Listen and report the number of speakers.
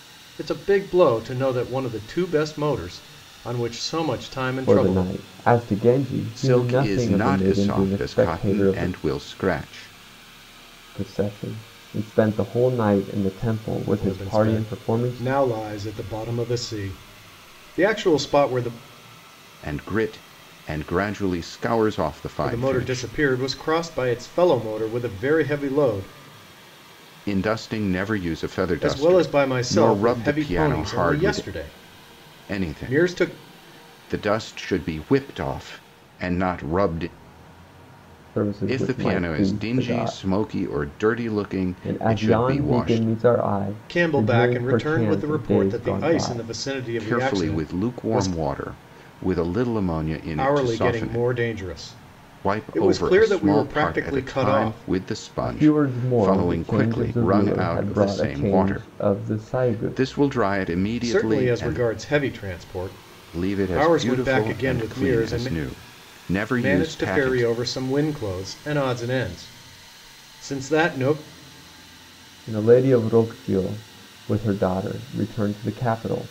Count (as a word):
three